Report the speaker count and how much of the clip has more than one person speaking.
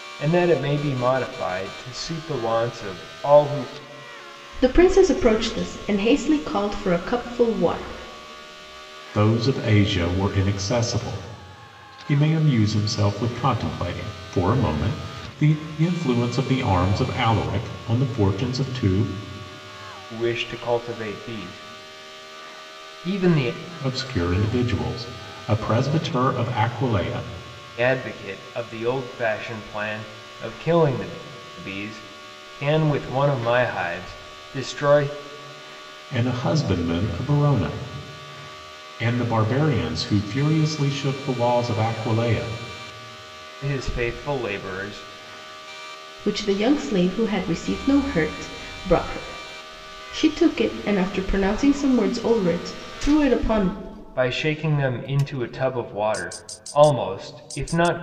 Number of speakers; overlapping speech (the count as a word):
three, no overlap